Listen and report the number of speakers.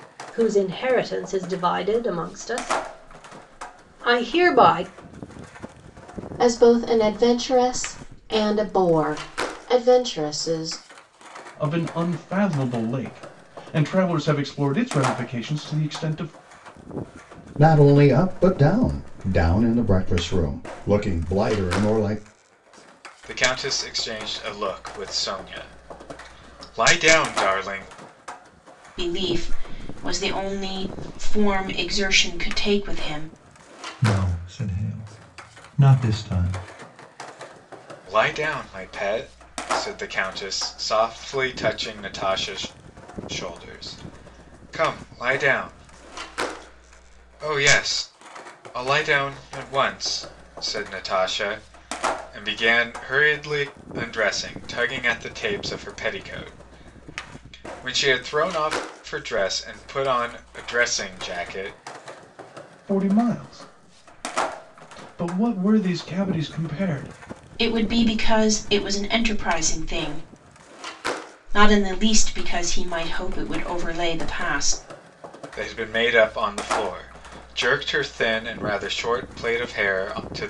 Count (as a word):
seven